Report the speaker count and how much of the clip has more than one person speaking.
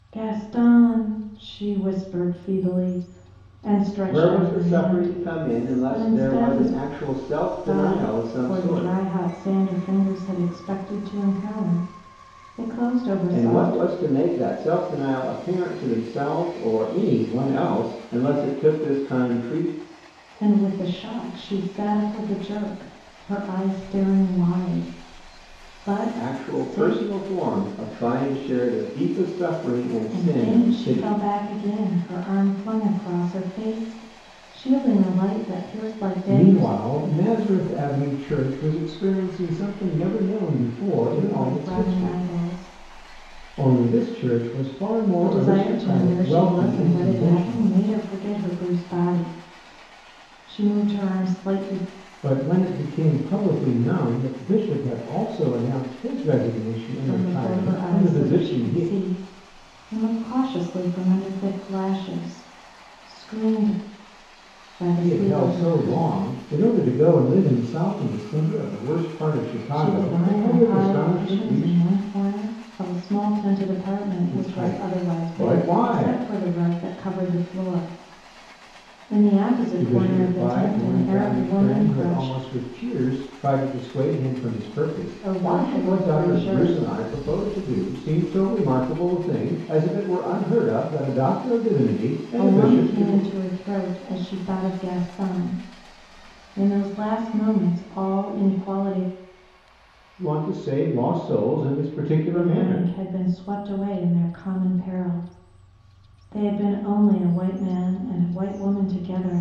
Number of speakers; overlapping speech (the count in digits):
2, about 22%